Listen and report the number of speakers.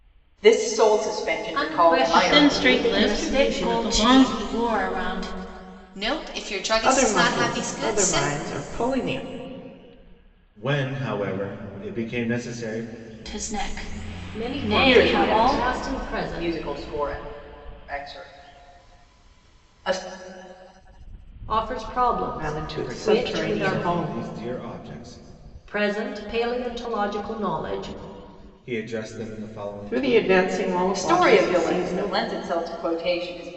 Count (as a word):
seven